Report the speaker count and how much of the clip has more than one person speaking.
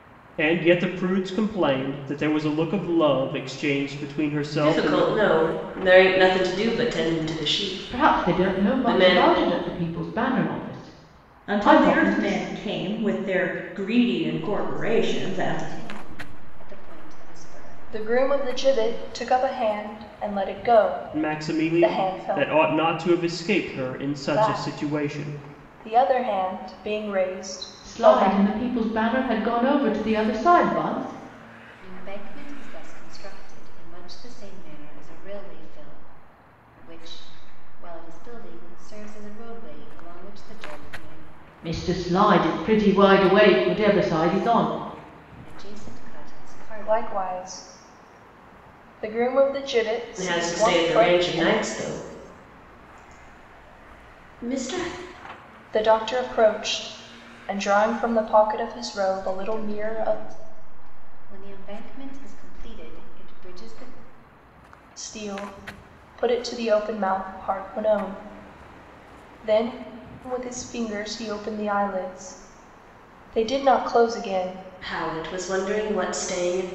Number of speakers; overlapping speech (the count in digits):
6, about 15%